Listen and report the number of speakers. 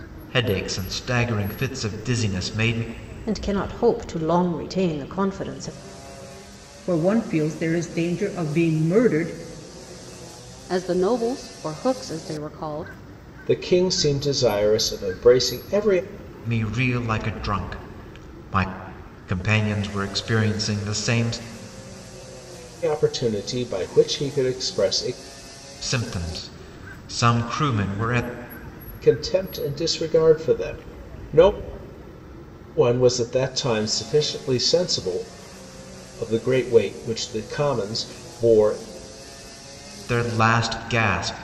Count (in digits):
5